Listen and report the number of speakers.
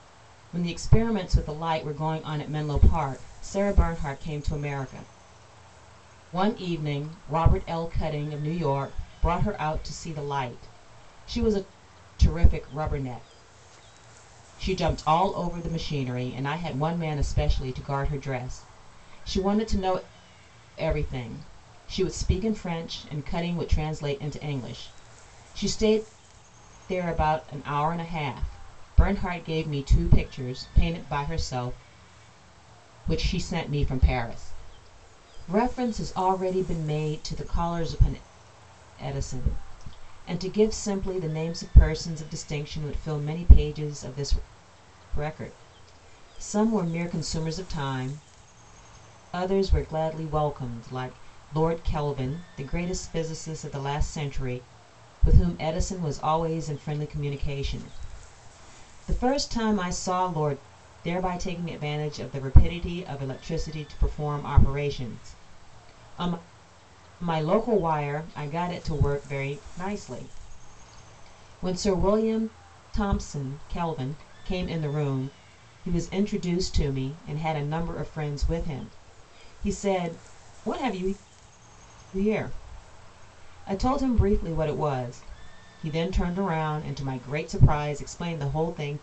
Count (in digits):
1